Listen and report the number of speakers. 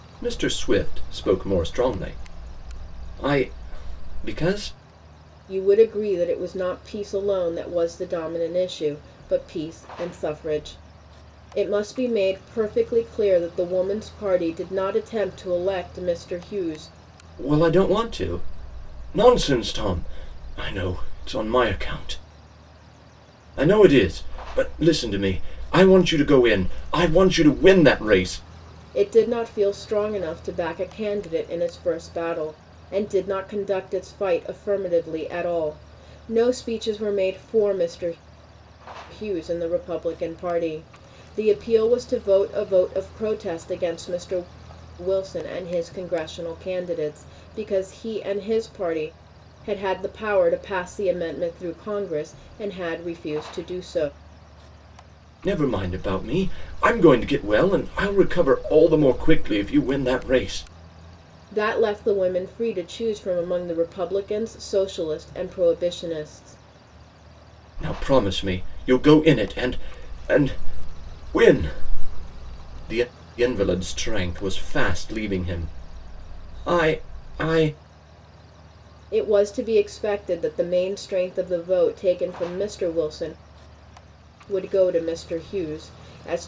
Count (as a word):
two